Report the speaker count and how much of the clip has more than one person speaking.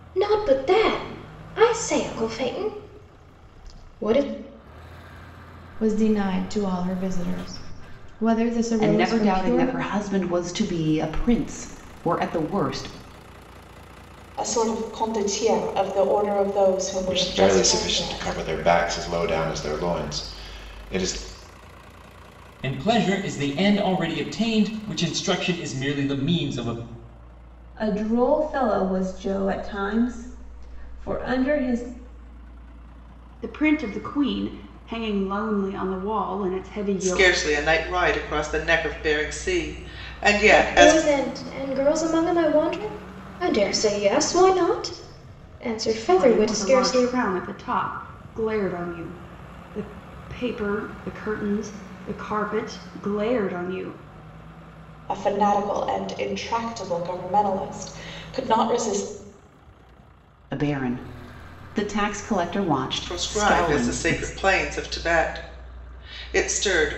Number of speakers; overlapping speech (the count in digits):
9, about 9%